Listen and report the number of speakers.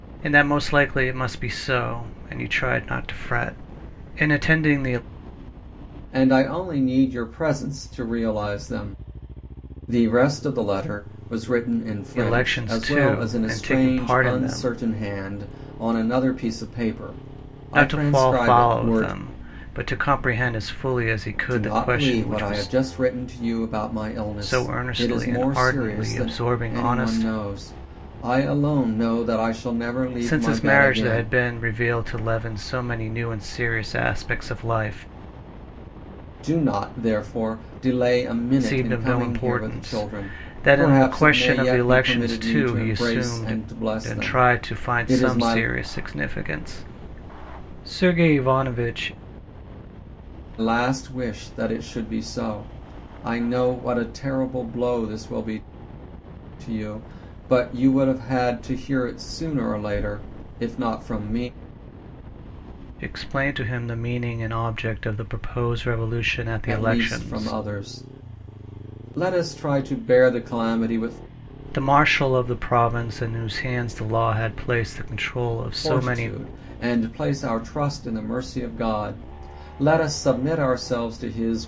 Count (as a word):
two